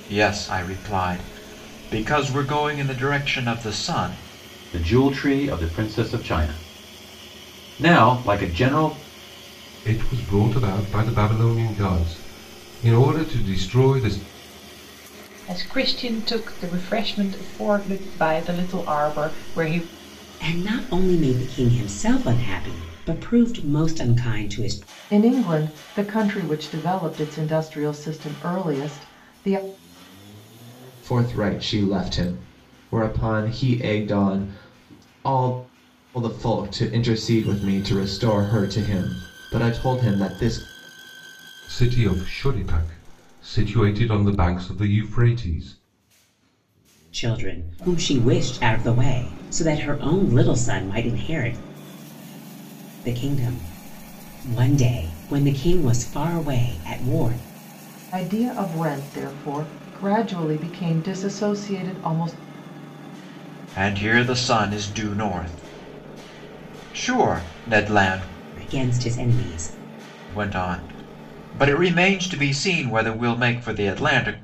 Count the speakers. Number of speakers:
7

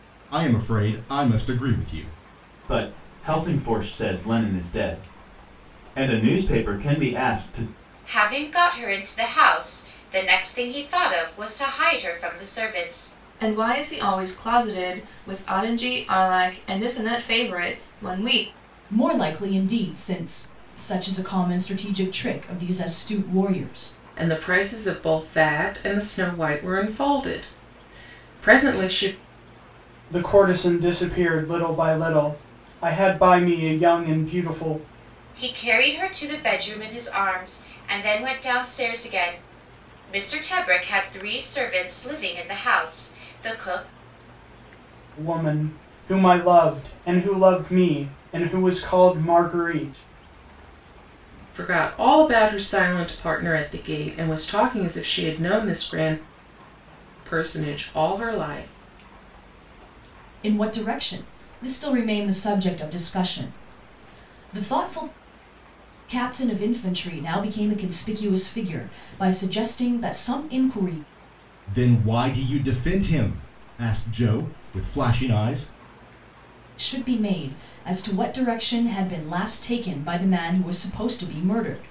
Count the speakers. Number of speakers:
7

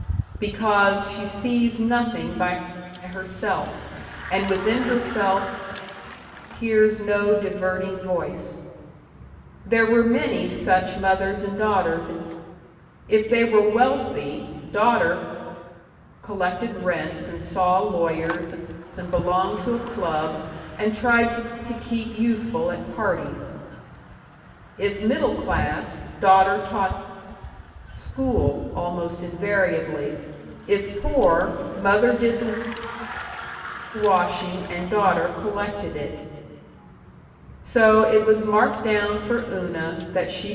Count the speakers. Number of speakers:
1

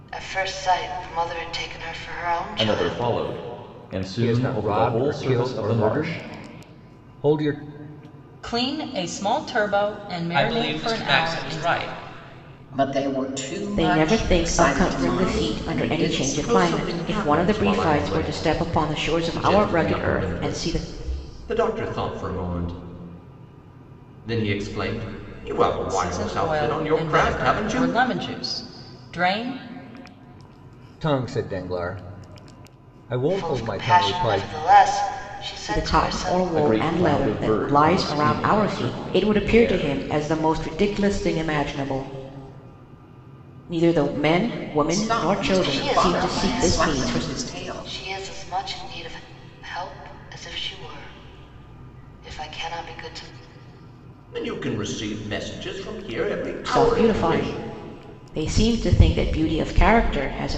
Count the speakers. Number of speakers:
8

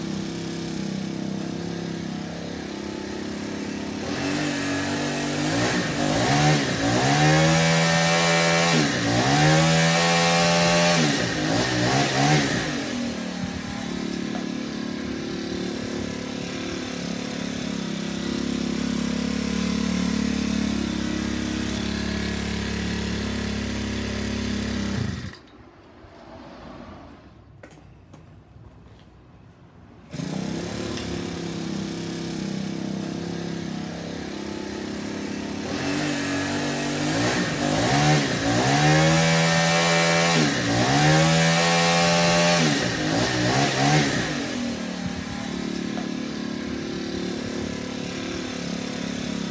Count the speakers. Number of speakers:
0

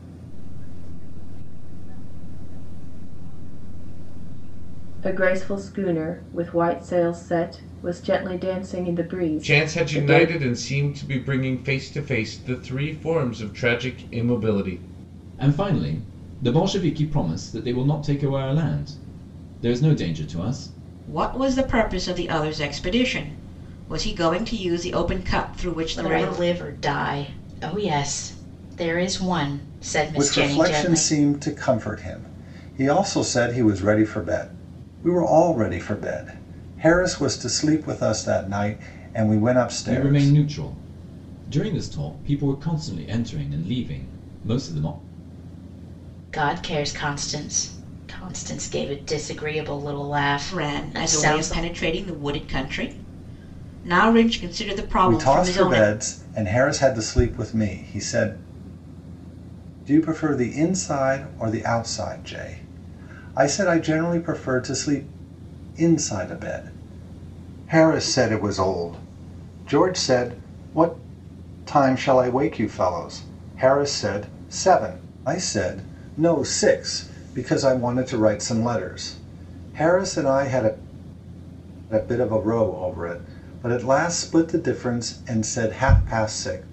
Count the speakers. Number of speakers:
7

